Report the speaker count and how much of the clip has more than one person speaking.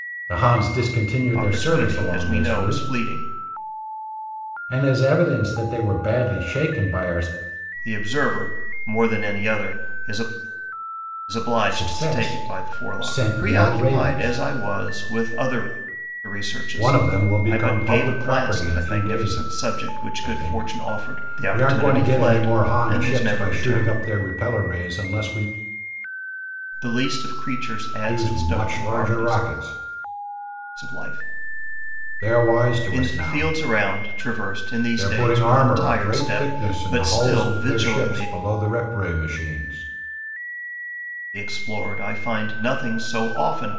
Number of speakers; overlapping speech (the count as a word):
two, about 38%